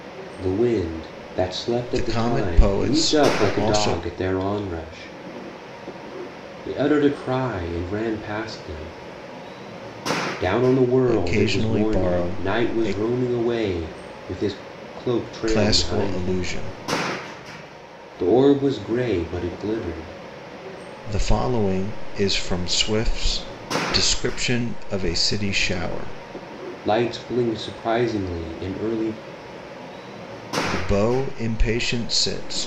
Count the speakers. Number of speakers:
2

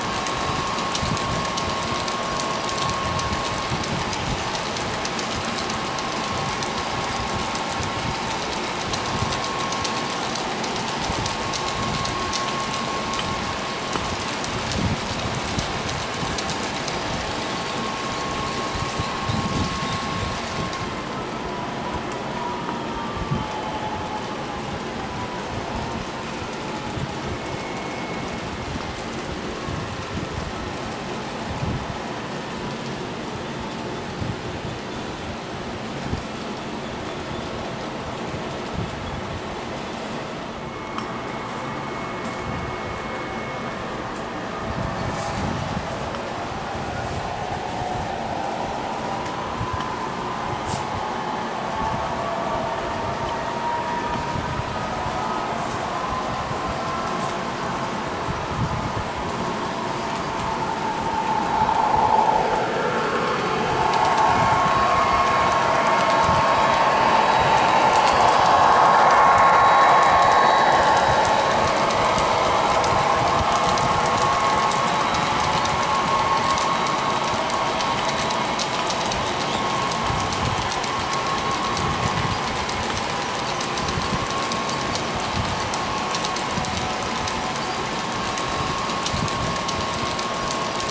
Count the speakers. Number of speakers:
0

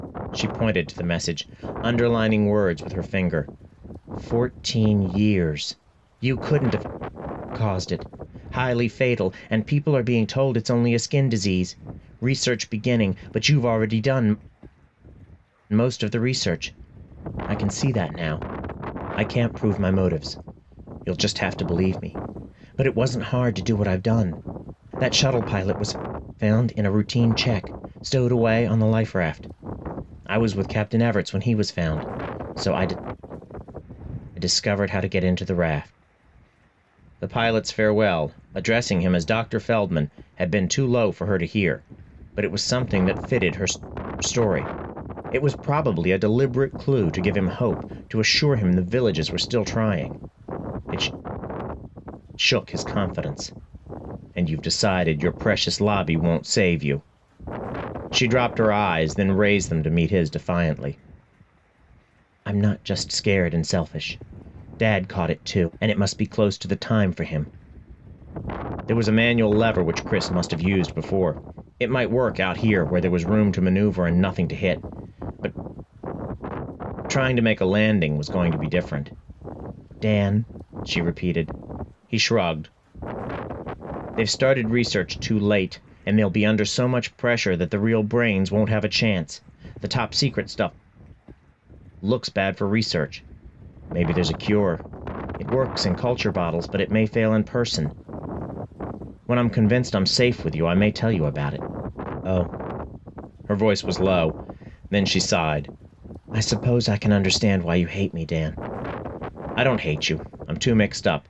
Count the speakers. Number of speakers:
1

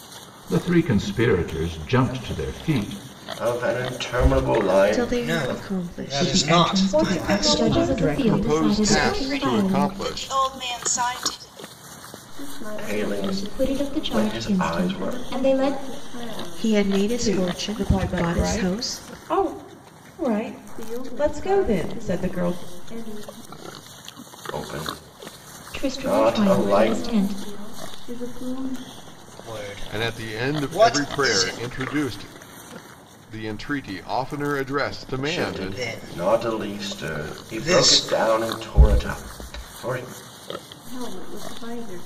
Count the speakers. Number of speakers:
10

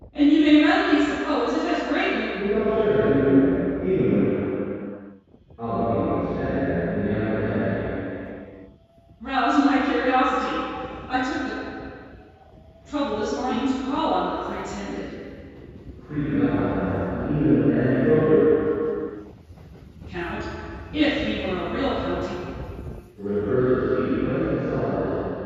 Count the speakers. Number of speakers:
2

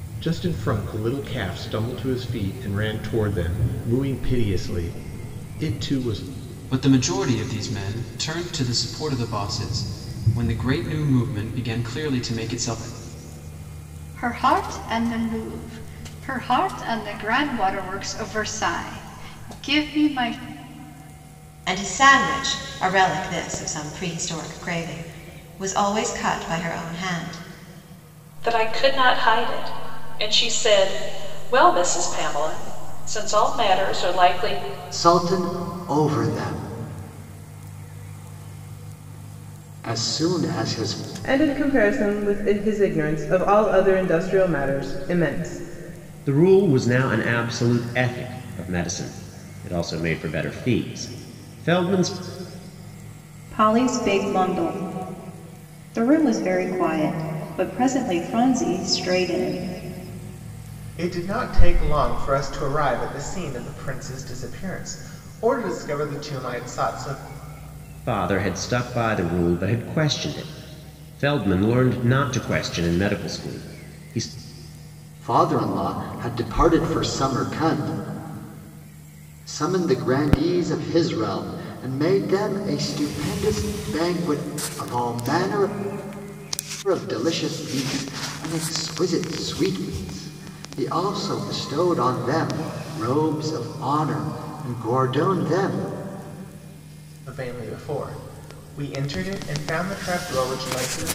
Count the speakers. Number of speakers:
10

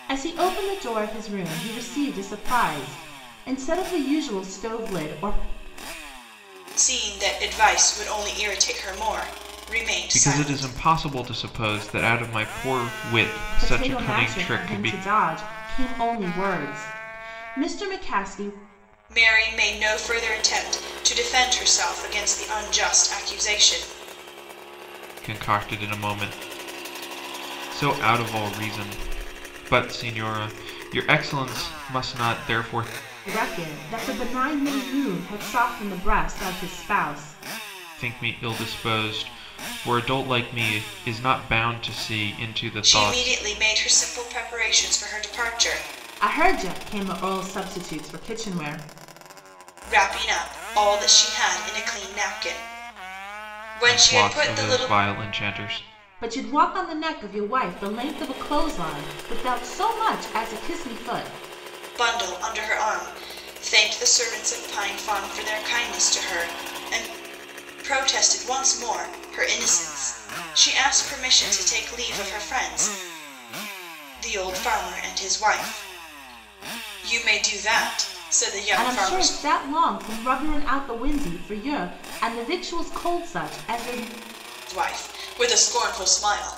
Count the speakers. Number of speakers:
3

